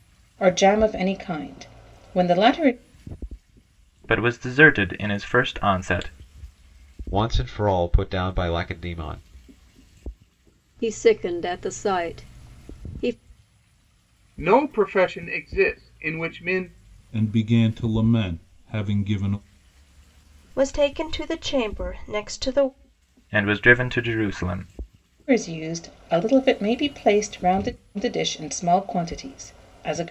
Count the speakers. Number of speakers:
seven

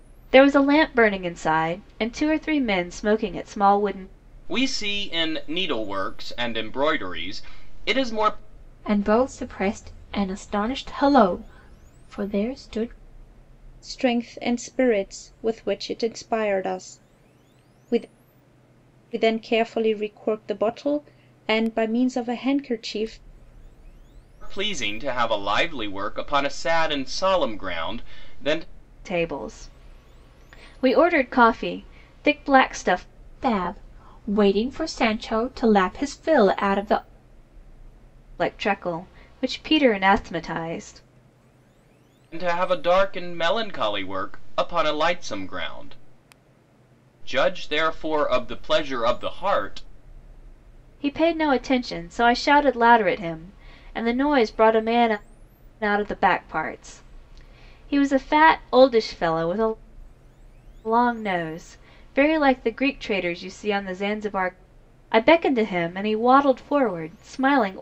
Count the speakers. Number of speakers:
four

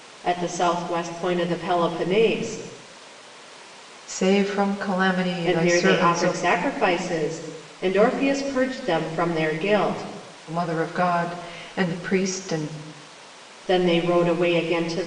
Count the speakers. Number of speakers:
two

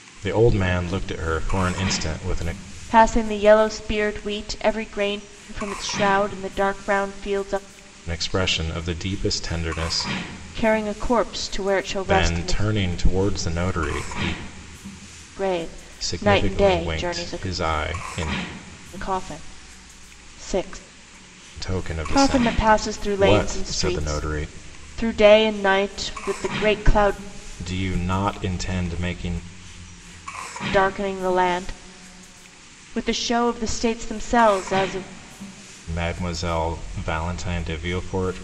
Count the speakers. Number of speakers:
two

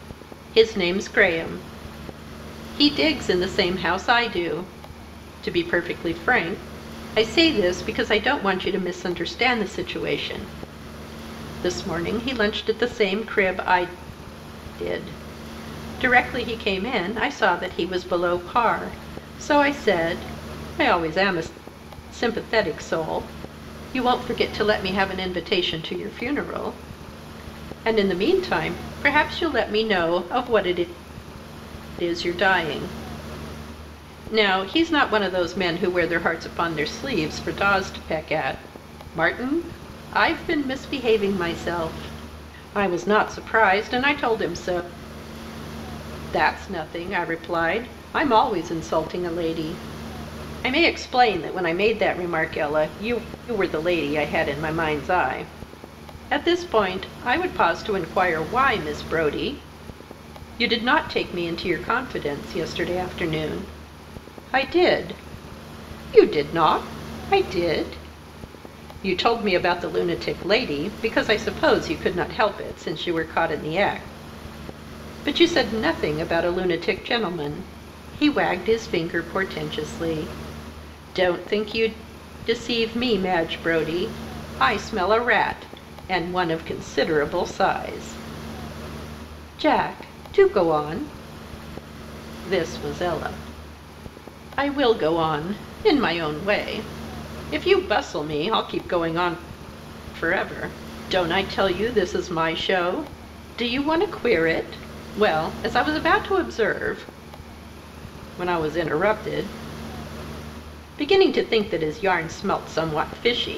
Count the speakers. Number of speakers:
one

